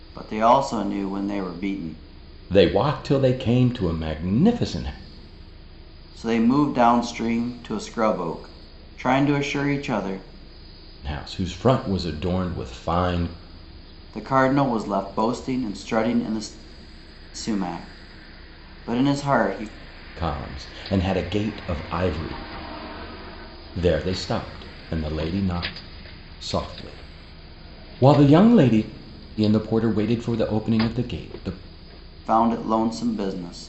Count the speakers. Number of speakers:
2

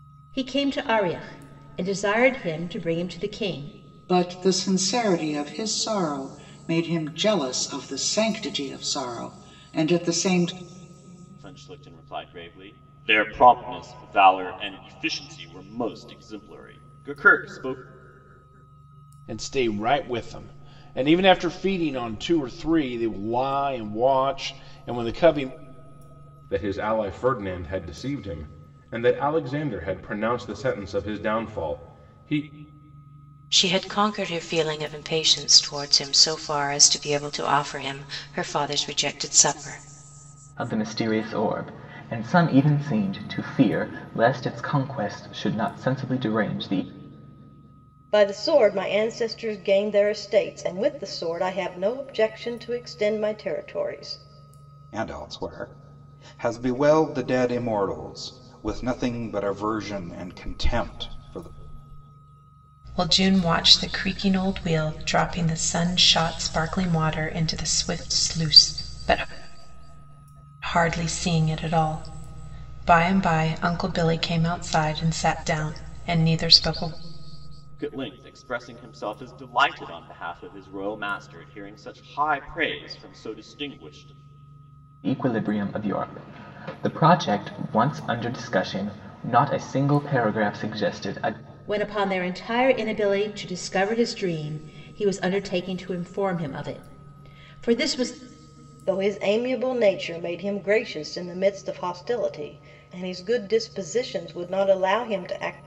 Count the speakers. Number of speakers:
10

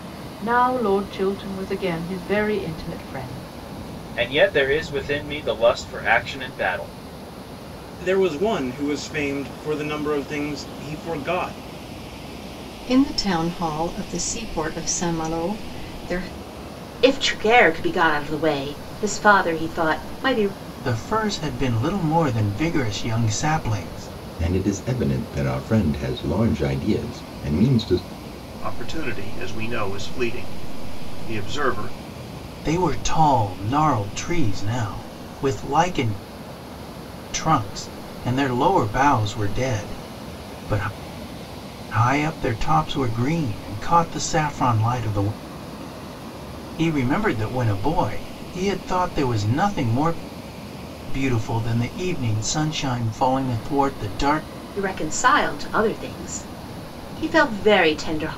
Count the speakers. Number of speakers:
8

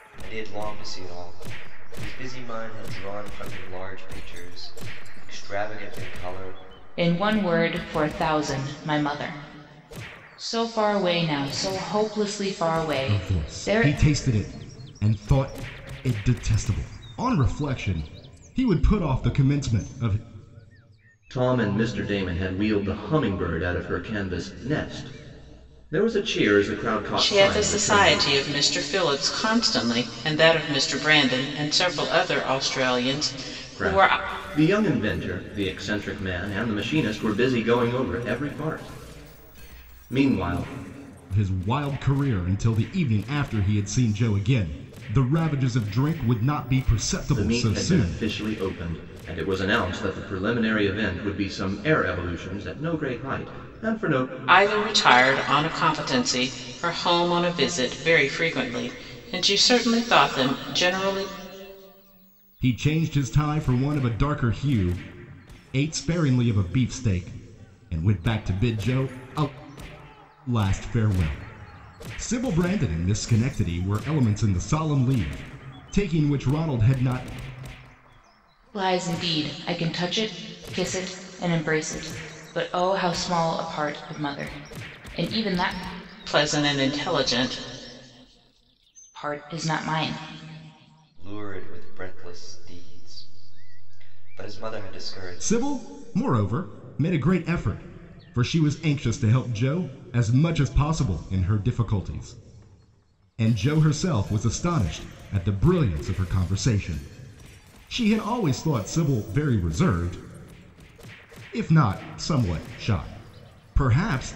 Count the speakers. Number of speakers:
5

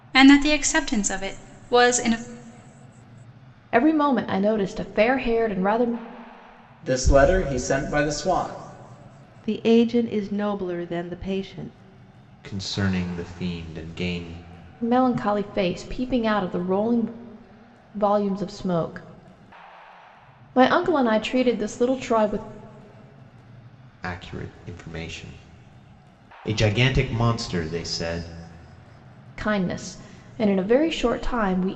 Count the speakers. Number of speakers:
5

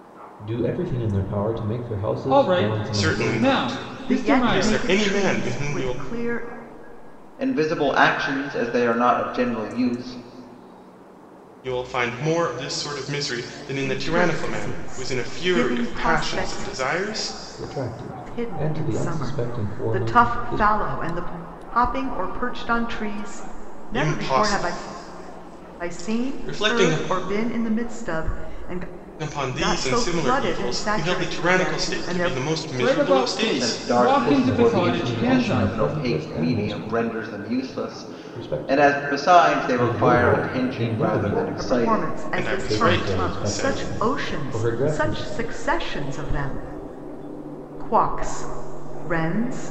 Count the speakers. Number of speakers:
5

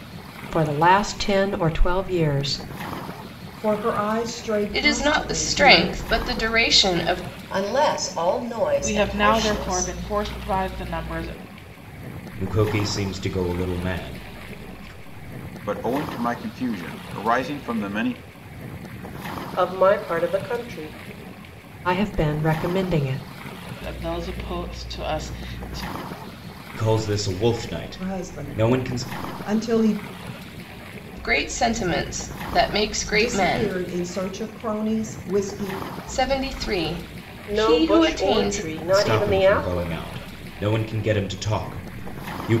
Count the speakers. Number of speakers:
8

